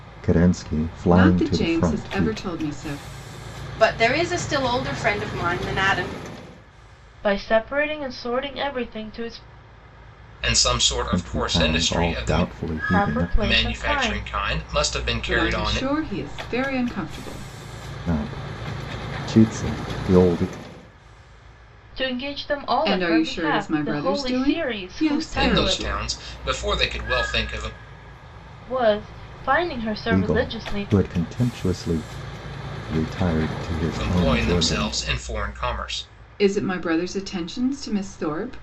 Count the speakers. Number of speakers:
5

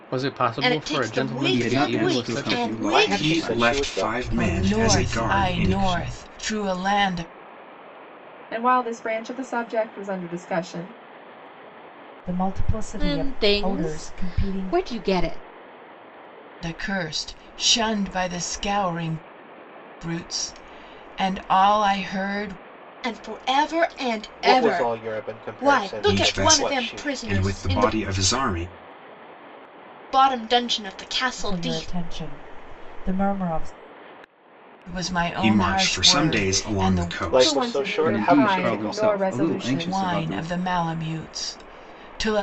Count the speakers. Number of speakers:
10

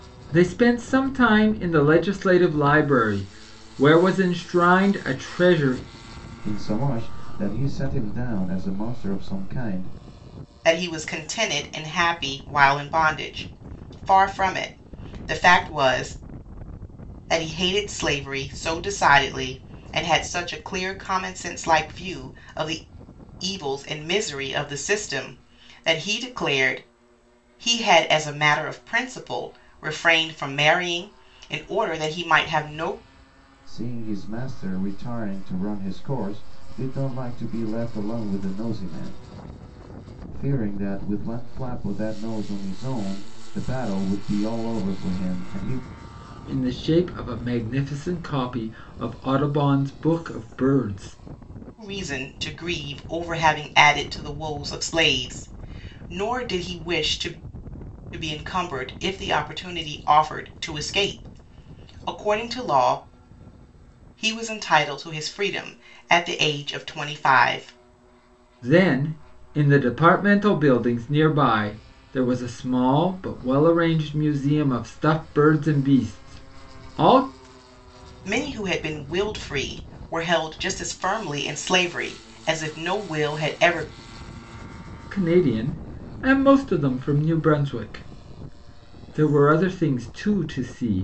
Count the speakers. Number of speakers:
3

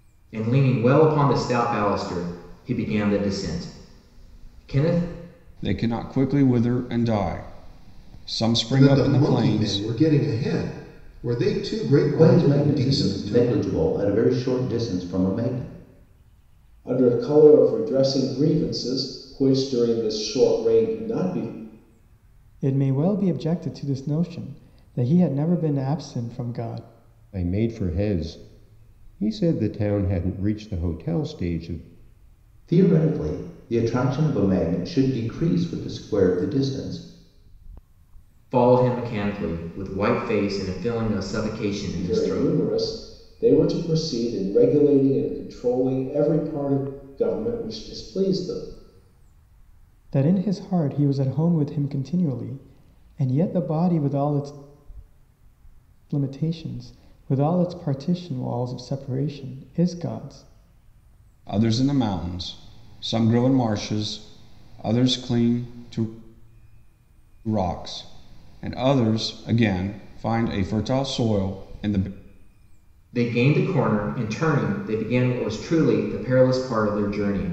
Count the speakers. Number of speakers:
7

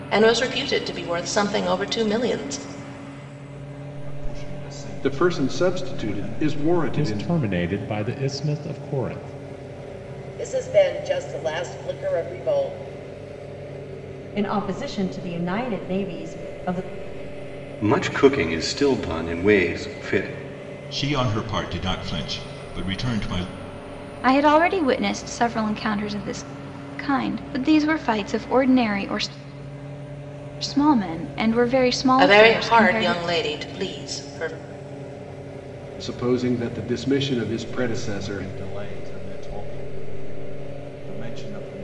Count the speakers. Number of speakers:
9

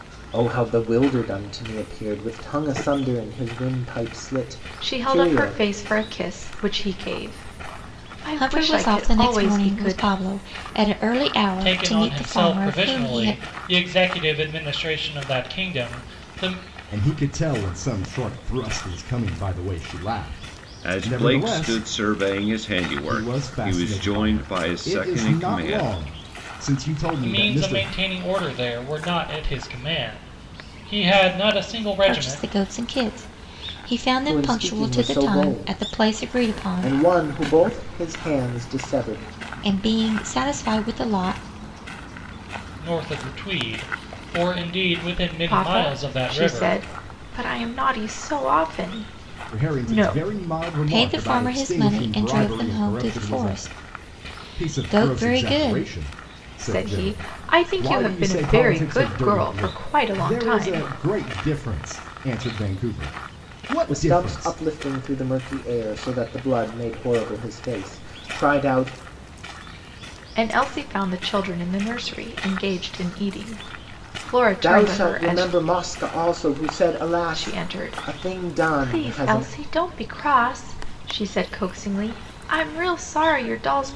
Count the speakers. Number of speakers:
6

